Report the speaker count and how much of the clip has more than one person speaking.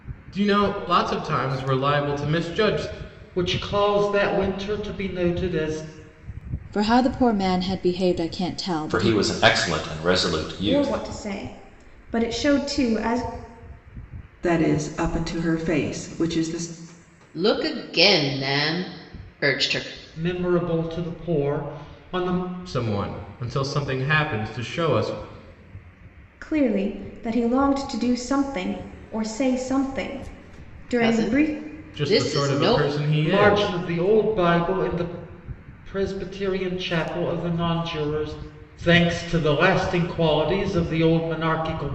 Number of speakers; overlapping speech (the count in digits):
7, about 7%